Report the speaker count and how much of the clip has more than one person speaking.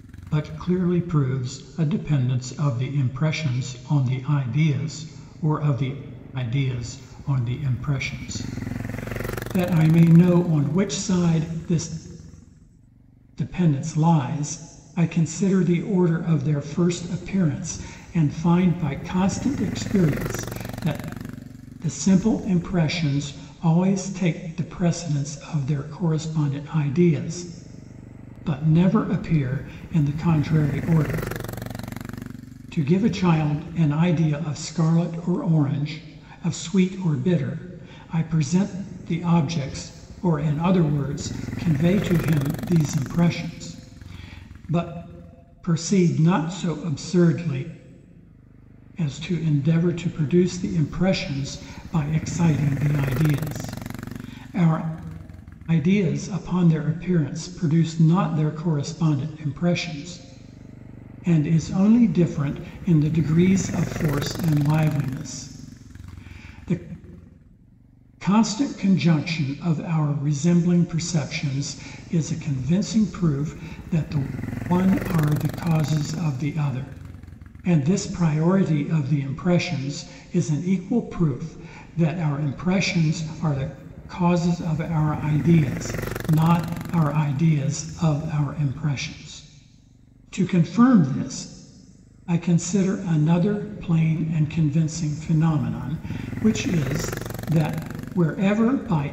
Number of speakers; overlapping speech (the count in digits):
1, no overlap